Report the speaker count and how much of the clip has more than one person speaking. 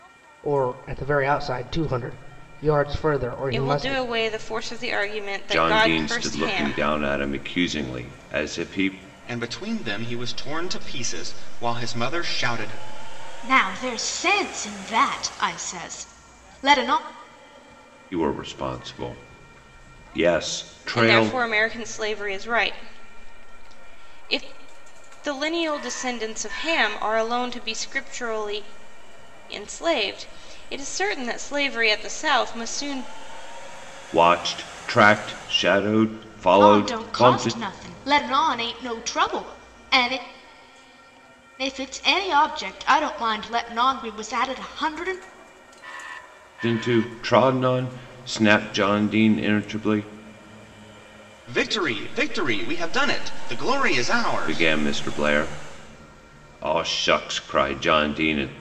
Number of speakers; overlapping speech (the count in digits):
5, about 6%